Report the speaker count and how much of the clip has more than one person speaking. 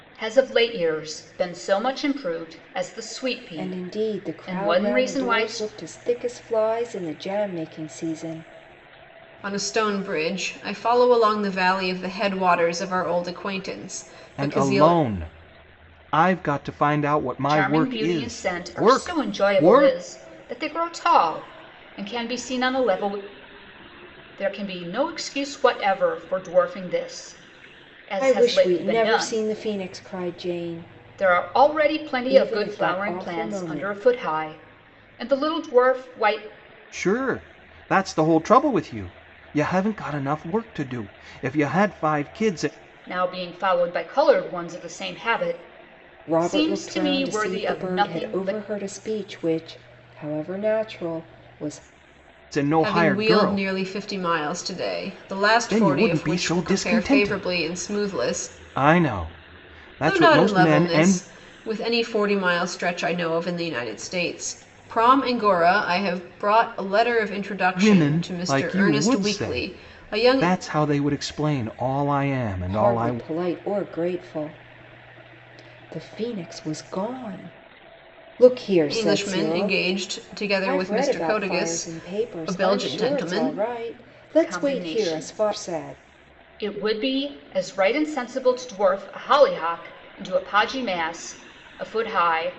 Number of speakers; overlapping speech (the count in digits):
4, about 28%